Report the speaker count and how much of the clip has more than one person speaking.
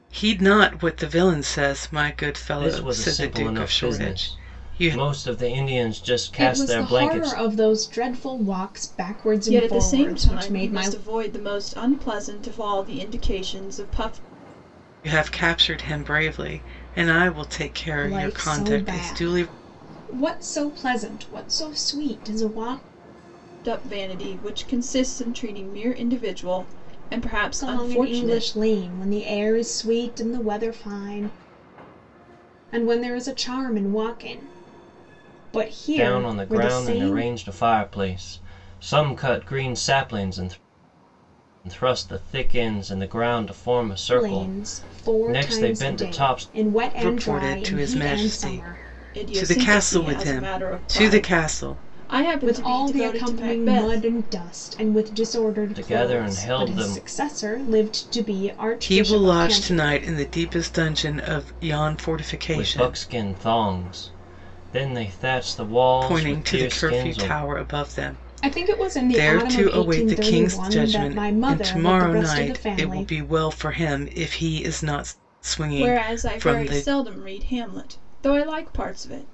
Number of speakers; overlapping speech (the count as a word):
four, about 35%